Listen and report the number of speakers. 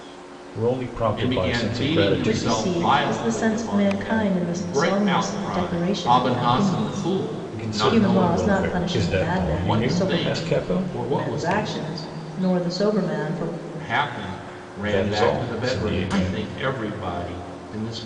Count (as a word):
three